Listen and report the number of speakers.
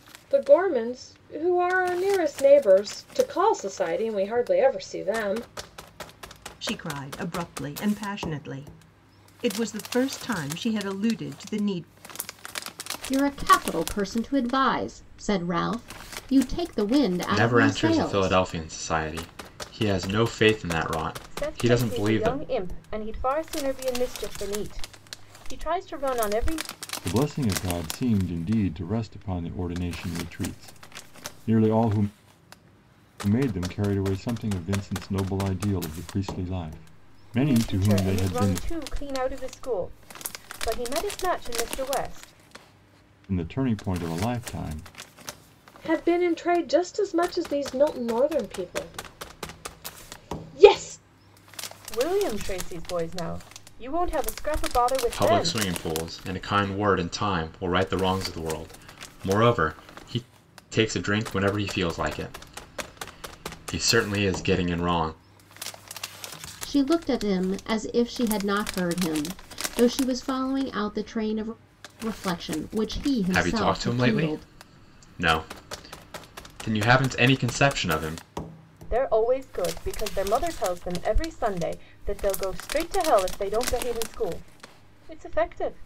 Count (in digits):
6